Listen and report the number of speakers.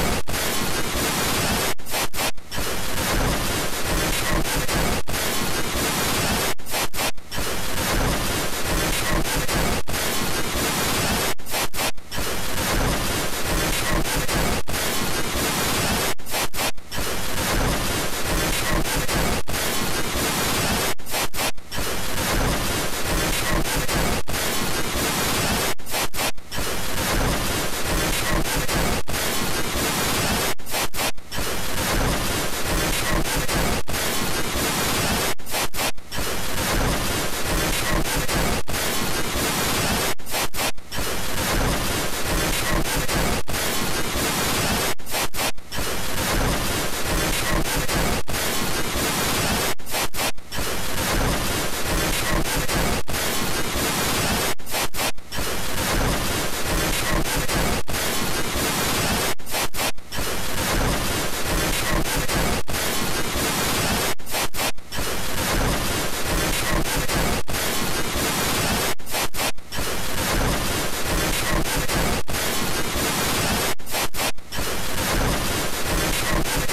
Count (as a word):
zero